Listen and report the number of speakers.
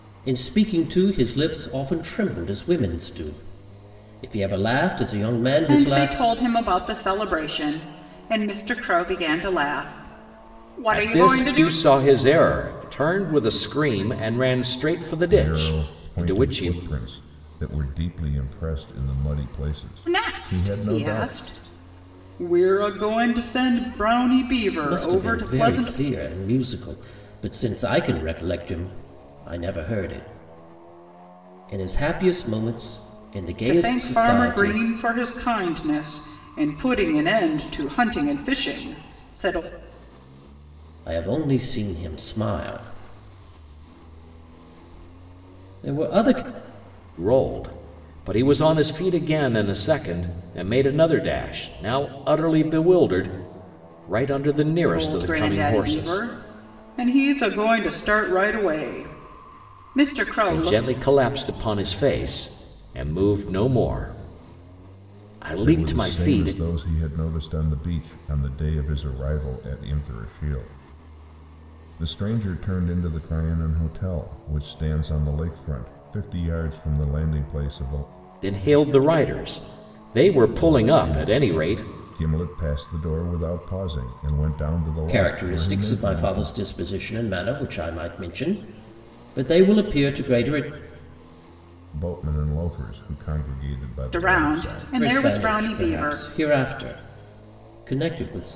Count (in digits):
4